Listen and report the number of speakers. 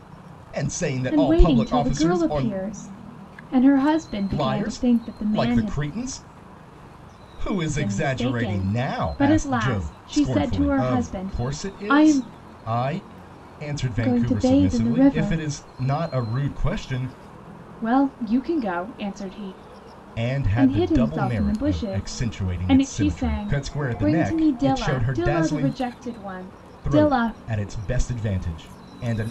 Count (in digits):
2